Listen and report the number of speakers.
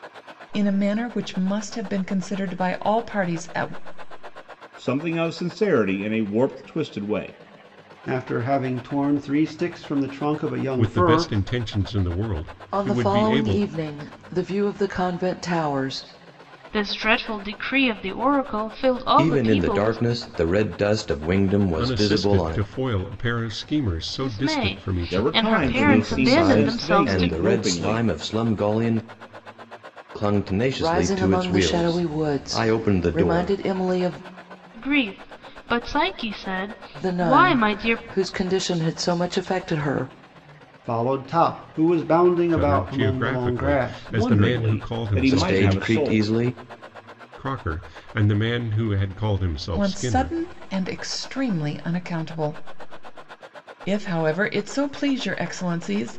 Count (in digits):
7